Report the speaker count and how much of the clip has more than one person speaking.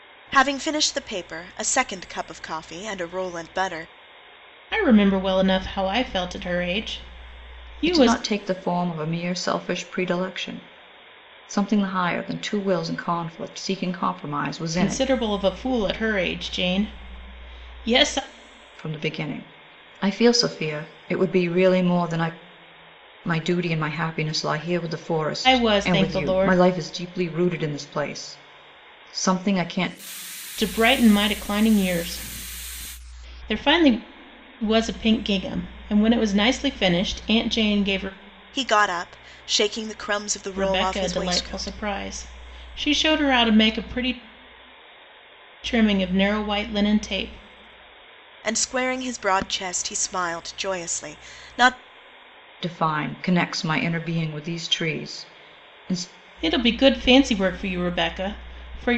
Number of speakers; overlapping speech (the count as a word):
three, about 5%